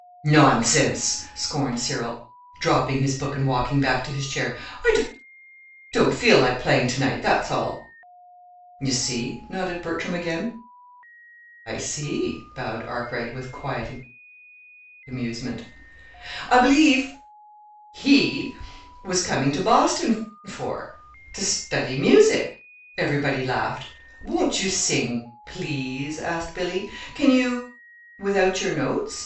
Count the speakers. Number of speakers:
1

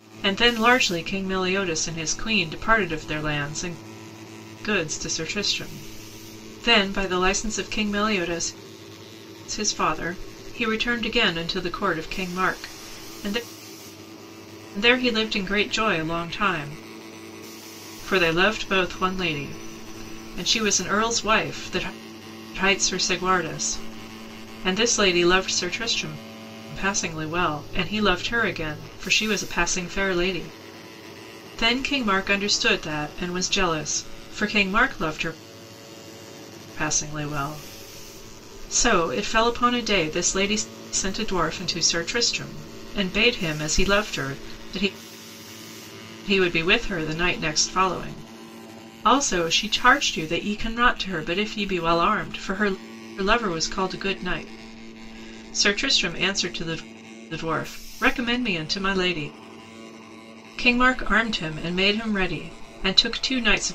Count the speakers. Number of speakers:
1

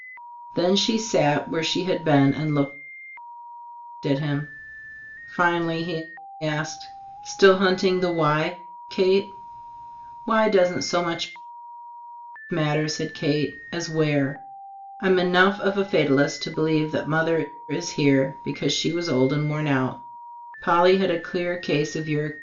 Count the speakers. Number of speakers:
1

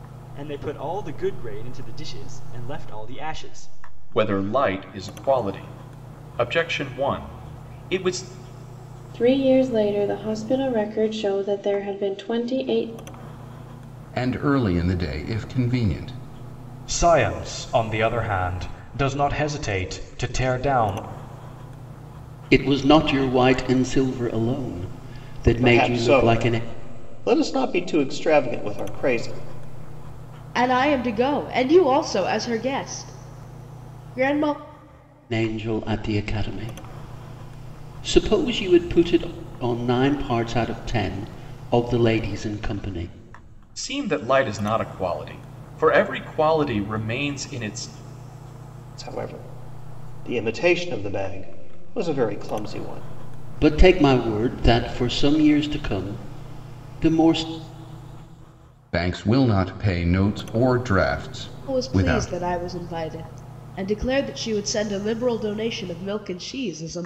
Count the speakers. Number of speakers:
8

